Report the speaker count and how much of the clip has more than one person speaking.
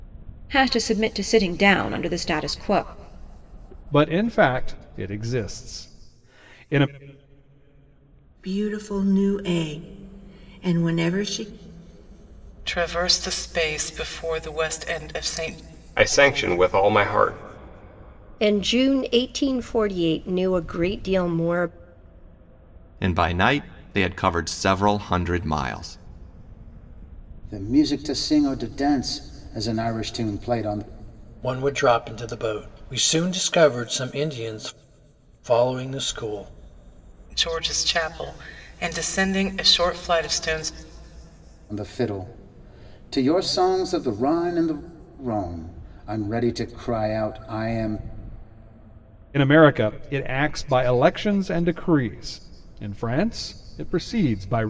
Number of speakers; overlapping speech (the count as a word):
nine, no overlap